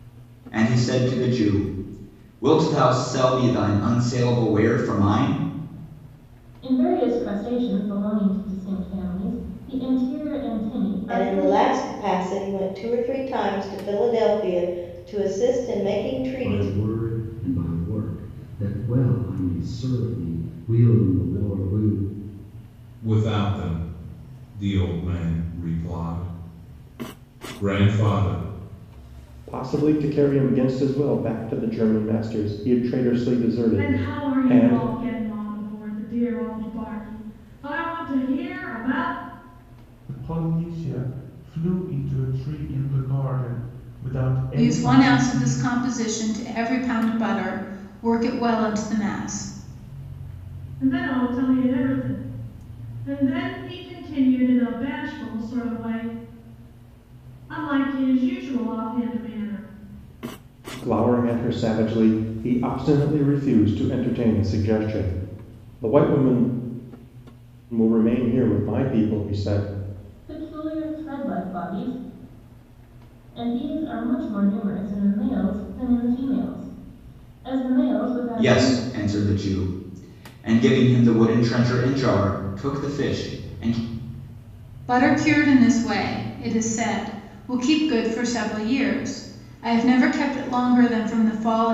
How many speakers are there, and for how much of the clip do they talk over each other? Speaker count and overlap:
nine, about 4%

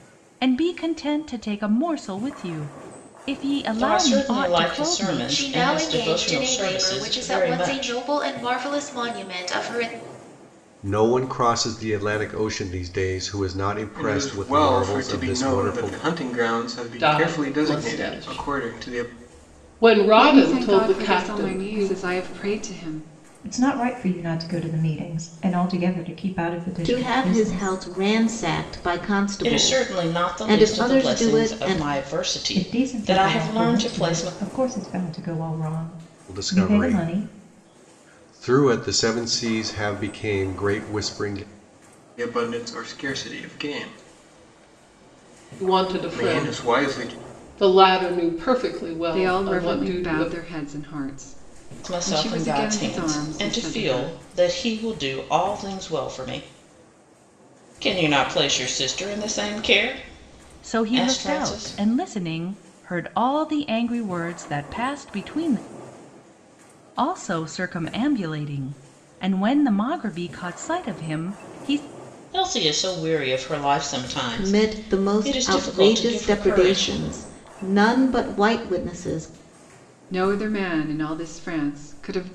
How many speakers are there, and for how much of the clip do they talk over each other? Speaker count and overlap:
nine, about 31%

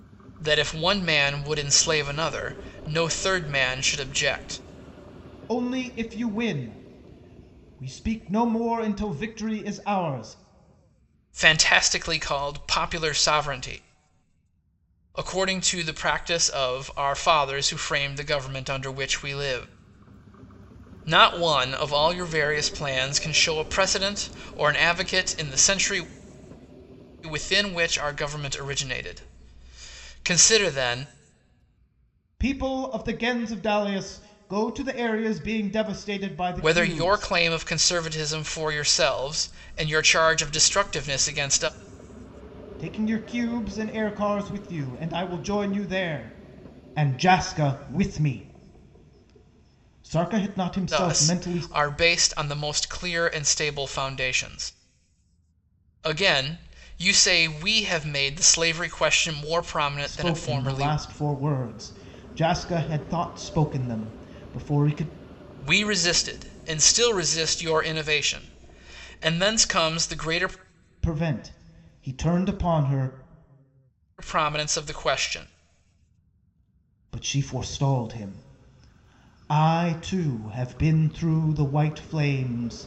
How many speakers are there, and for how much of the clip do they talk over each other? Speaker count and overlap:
two, about 3%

